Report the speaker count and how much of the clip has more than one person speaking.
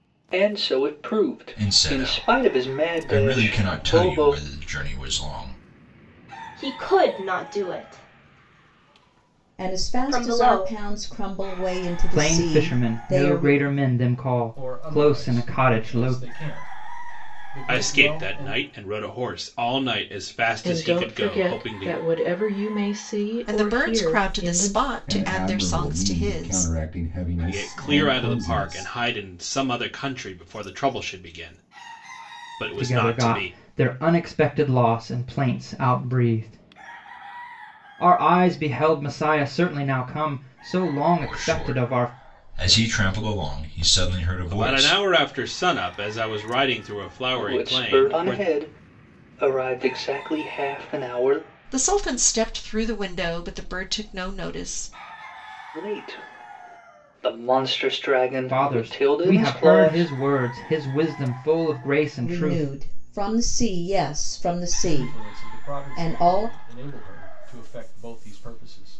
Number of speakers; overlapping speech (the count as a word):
ten, about 31%